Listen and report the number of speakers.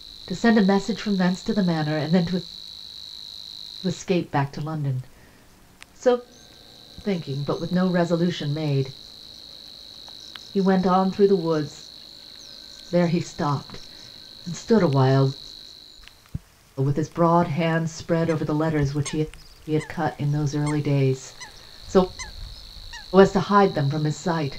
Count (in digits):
1